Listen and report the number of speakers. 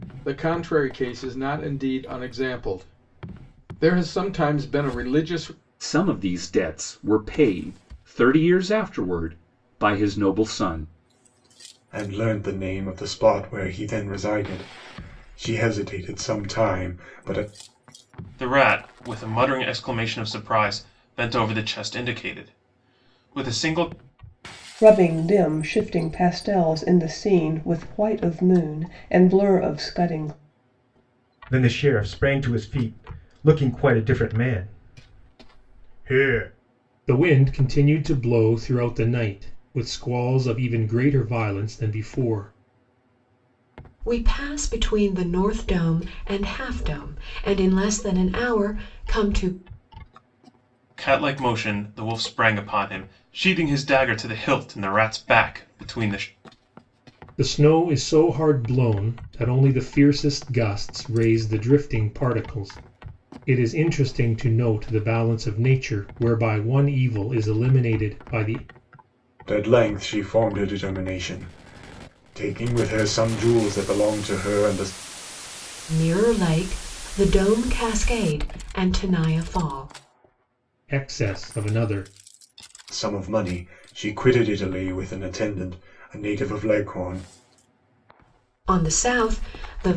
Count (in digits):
8